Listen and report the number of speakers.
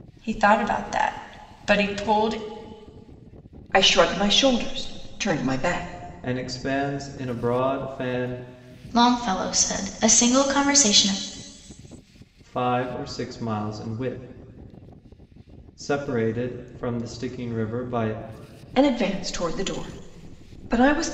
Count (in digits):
4